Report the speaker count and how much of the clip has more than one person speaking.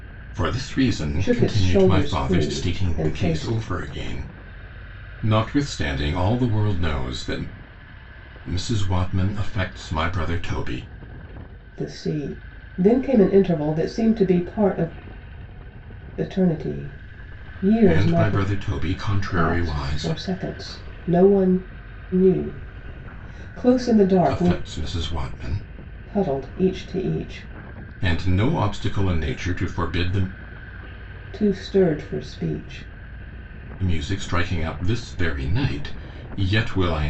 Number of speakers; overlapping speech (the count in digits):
2, about 12%